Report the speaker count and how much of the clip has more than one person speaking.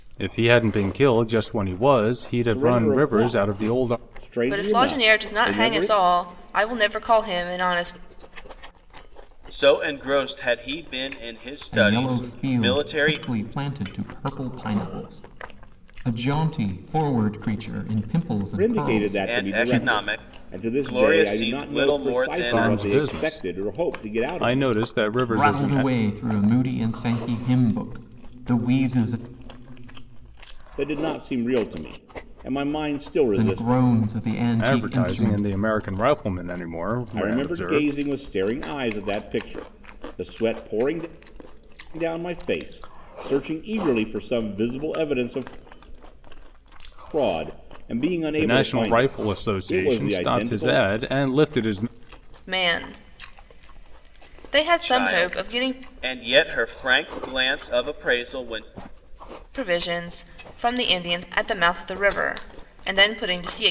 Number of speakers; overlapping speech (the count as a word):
five, about 27%